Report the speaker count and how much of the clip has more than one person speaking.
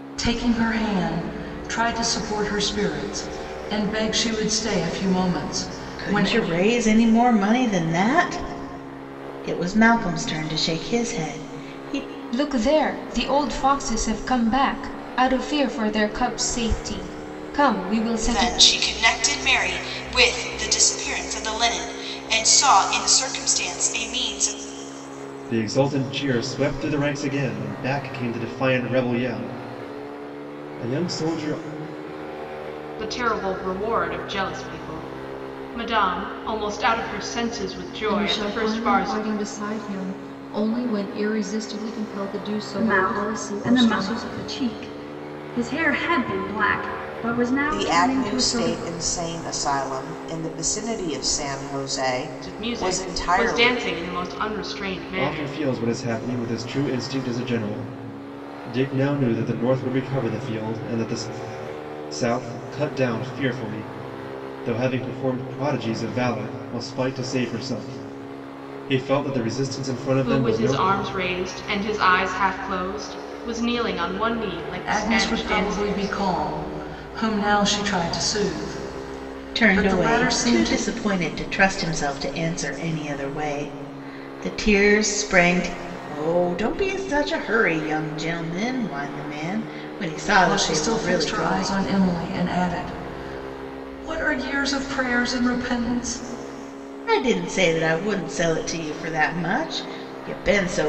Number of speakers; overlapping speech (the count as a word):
nine, about 11%